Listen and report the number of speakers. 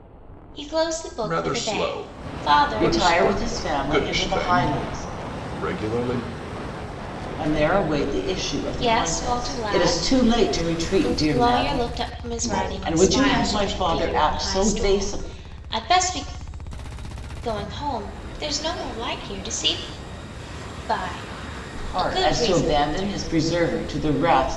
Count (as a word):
three